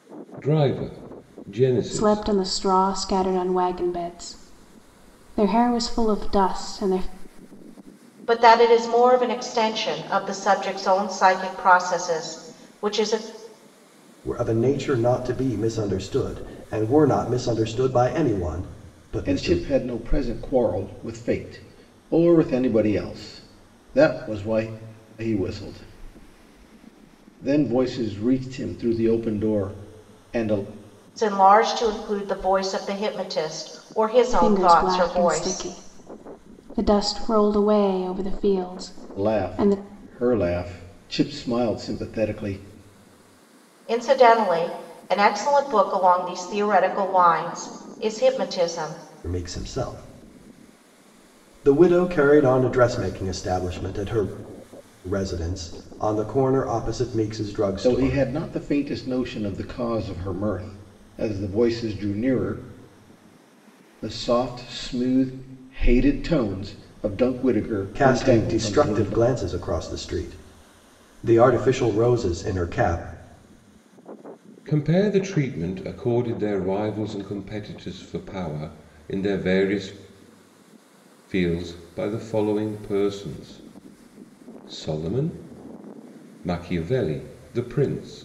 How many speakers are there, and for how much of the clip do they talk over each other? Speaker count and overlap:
5, about 5%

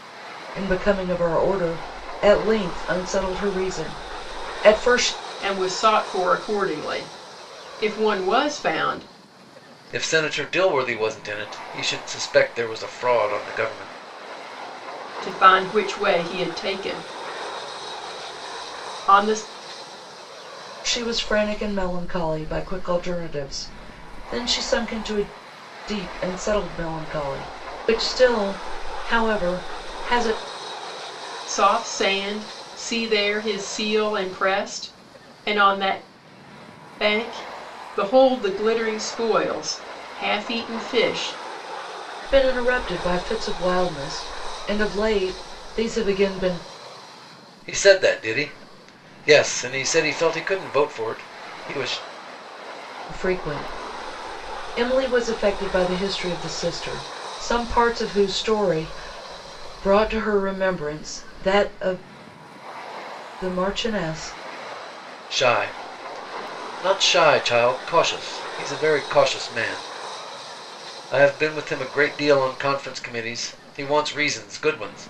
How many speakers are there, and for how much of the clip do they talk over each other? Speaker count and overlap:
3, no overlap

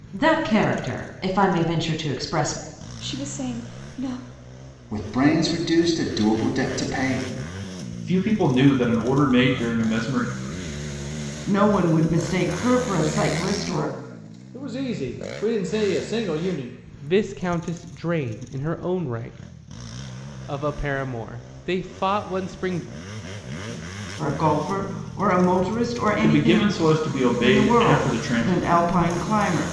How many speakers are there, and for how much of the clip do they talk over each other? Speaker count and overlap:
7, about 6%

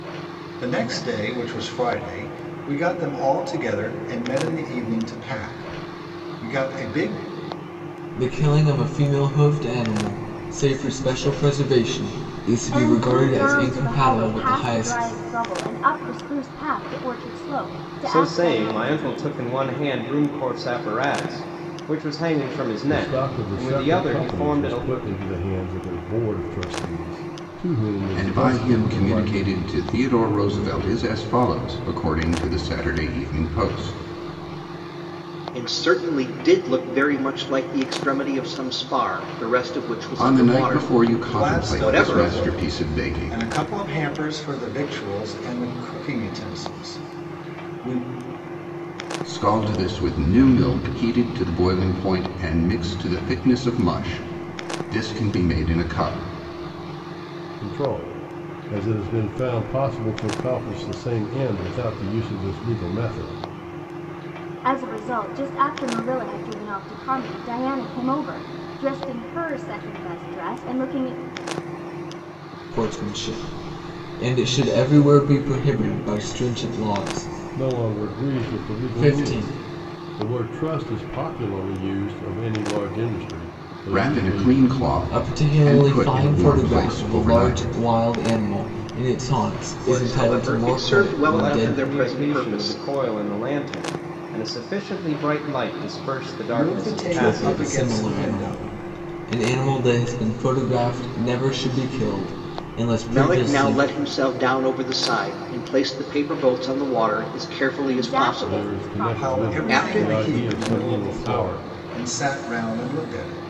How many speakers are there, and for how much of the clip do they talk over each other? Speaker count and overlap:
7, about 22%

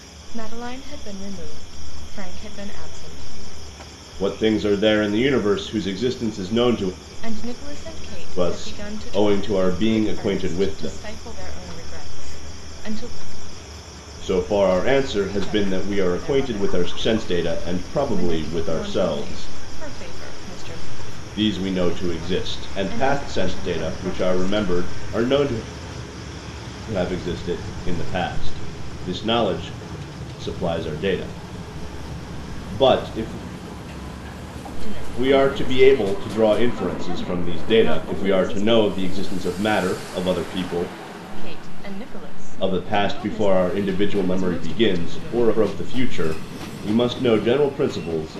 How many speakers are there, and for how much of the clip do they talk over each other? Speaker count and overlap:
2, about 36%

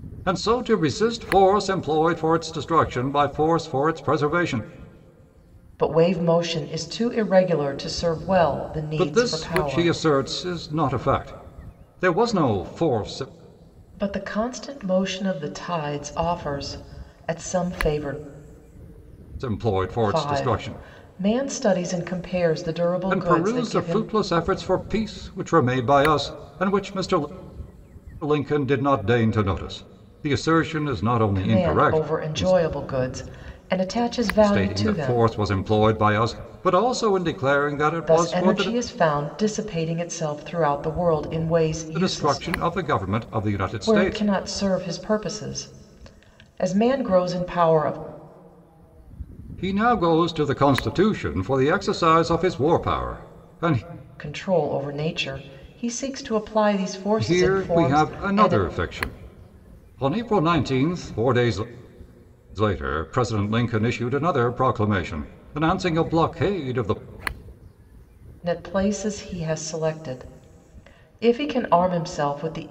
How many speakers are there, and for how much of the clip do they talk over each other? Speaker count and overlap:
2, about 11%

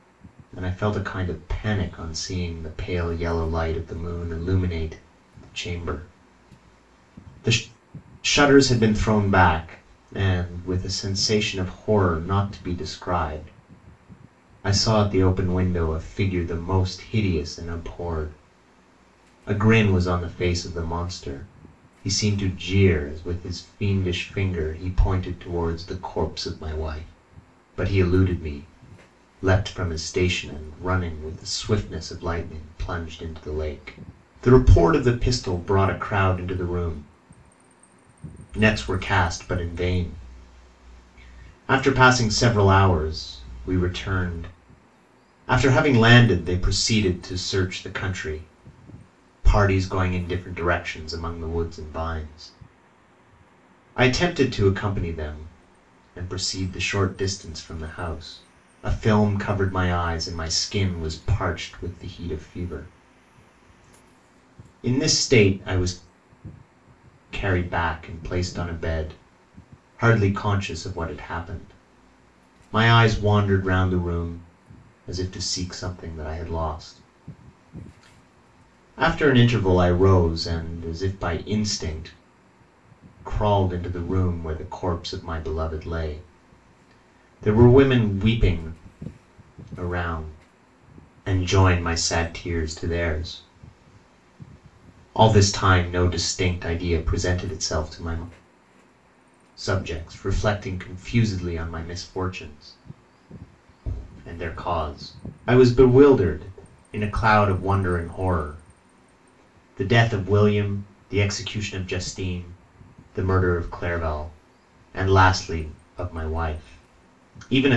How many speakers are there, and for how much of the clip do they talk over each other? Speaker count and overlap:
1, no overlap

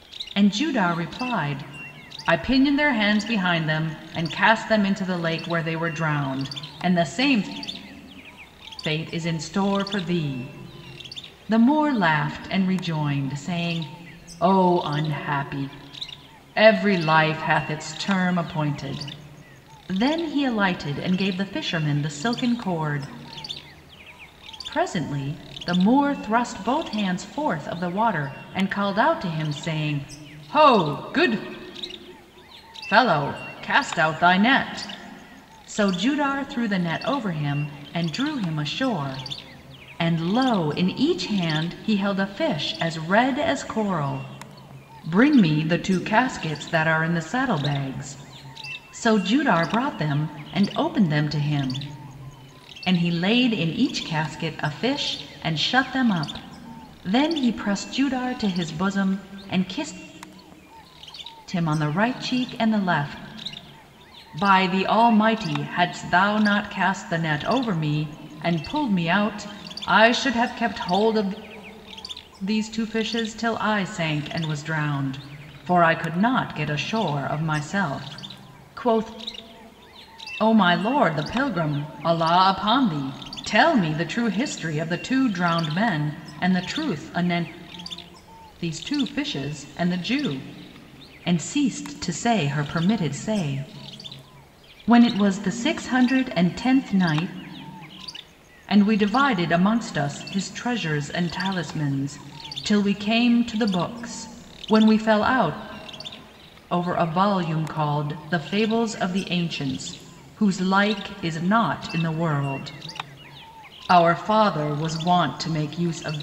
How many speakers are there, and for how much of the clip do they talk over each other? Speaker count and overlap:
1, no overlap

